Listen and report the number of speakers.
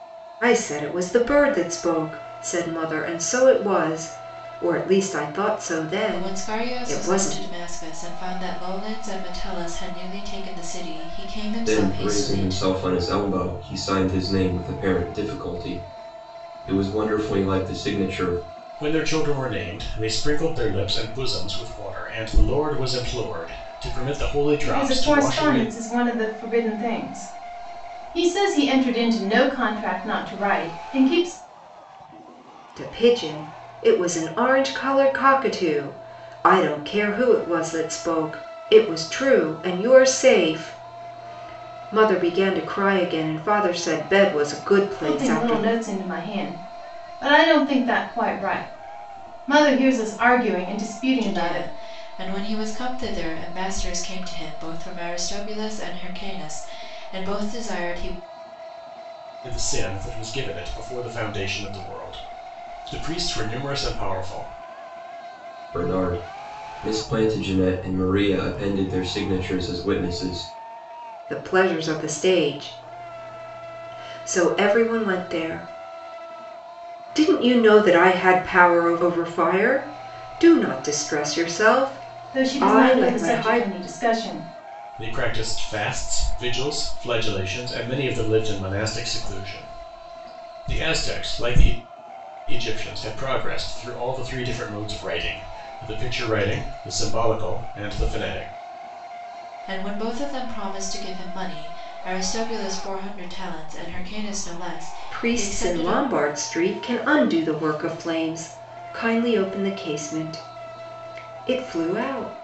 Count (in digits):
5